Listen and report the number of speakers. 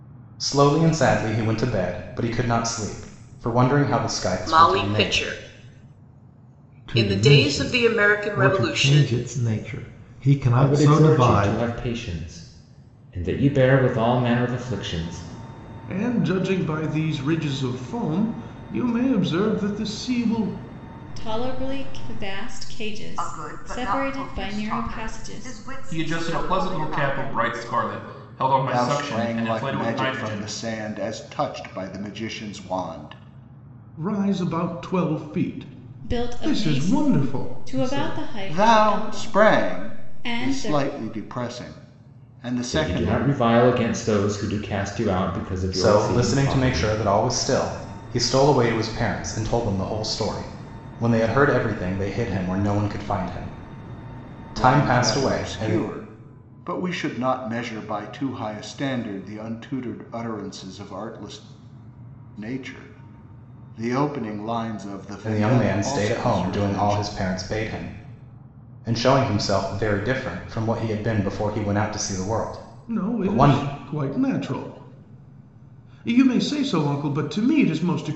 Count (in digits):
9